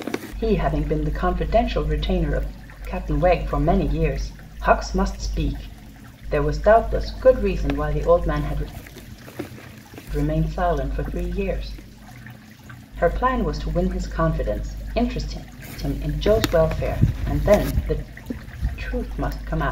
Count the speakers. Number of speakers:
1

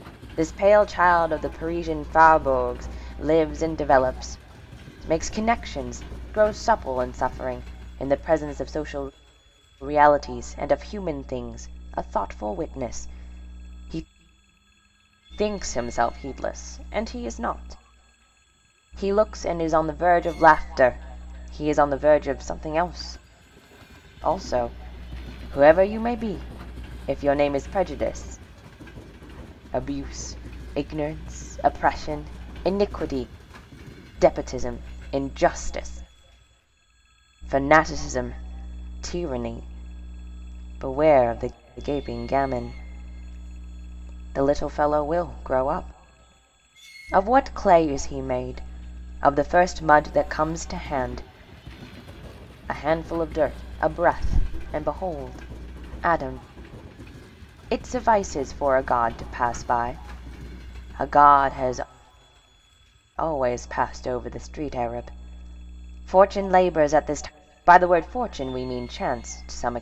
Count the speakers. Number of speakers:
1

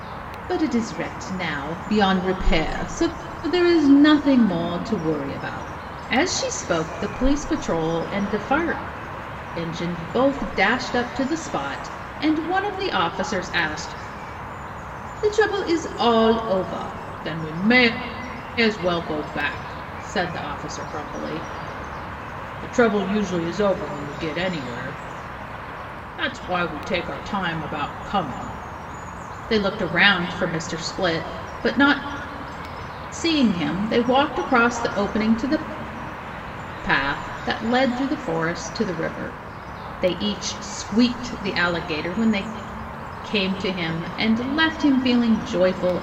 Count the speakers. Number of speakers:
1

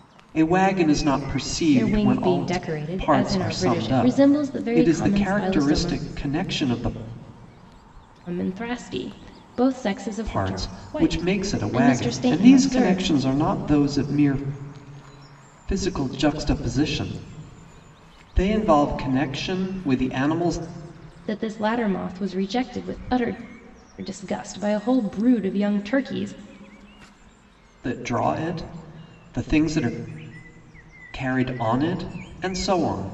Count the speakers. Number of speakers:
2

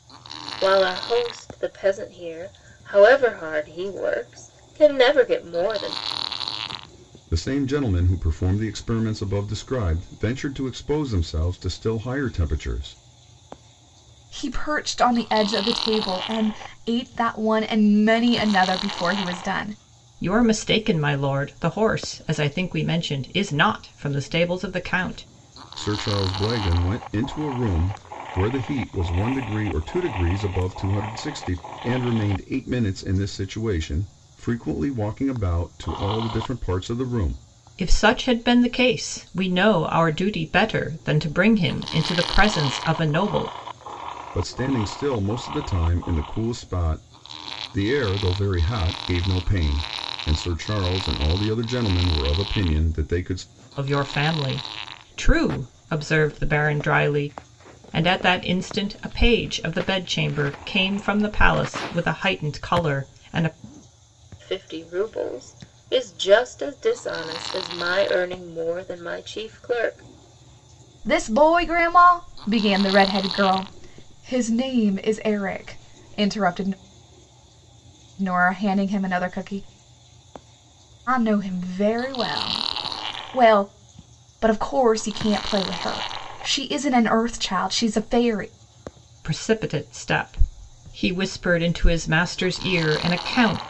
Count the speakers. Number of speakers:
4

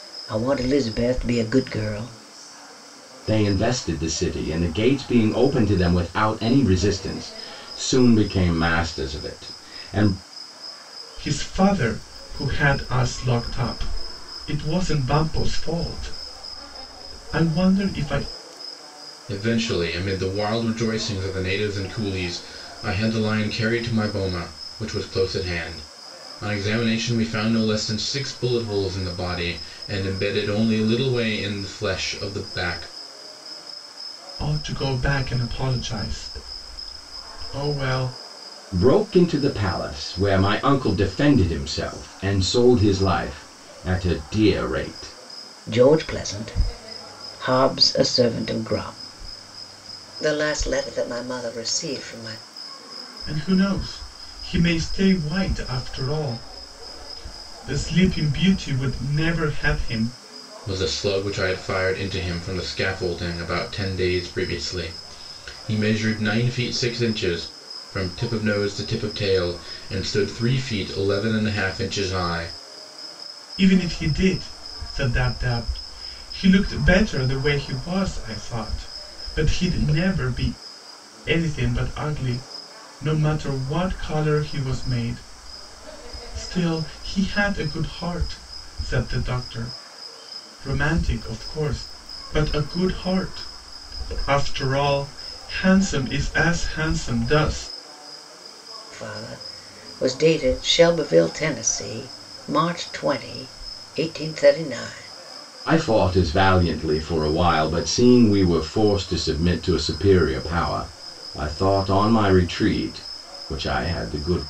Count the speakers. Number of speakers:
4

